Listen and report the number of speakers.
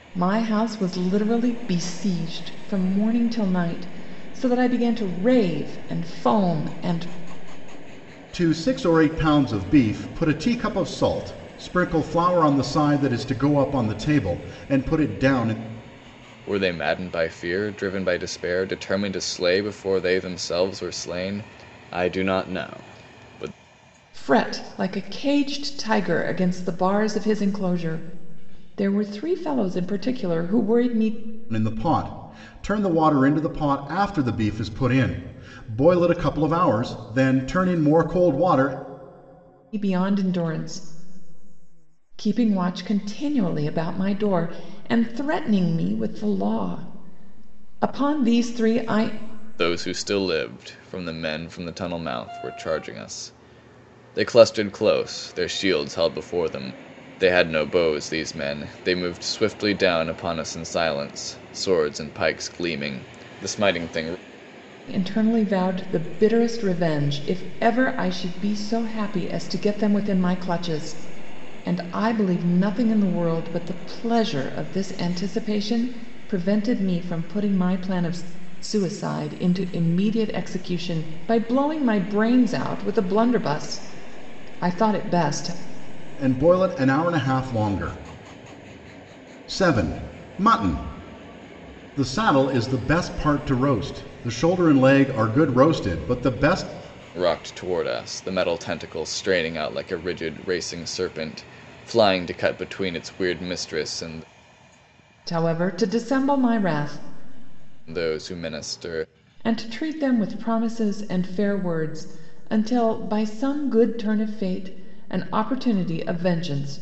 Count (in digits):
3